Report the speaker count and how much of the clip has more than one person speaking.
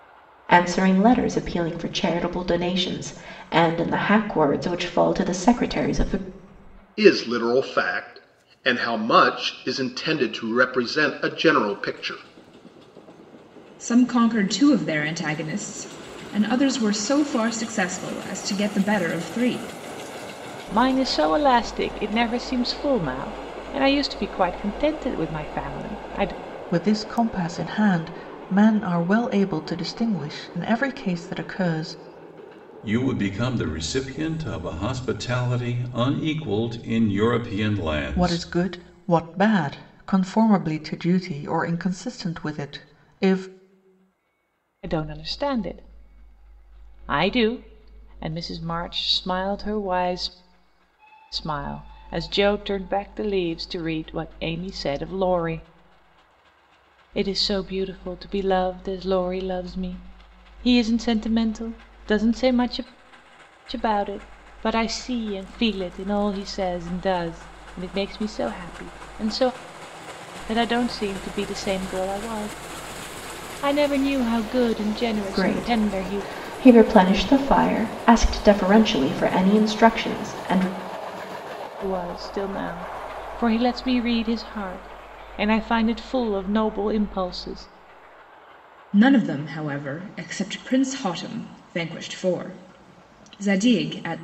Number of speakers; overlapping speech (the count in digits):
6, about 1%